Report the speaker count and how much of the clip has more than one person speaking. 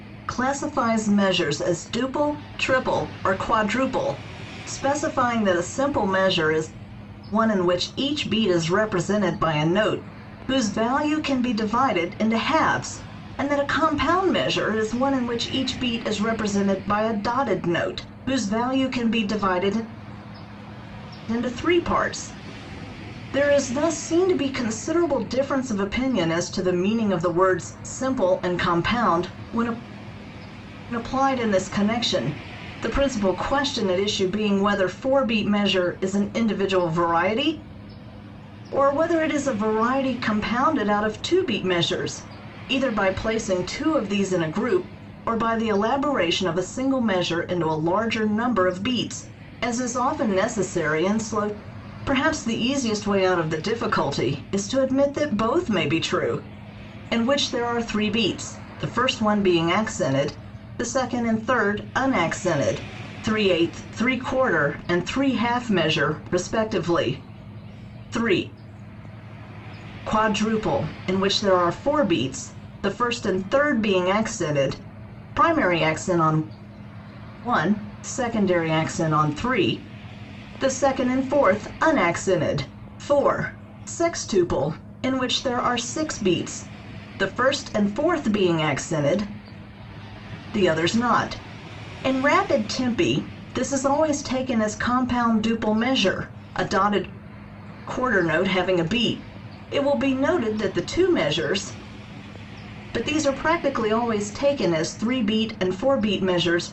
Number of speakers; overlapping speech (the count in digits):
1, no overlap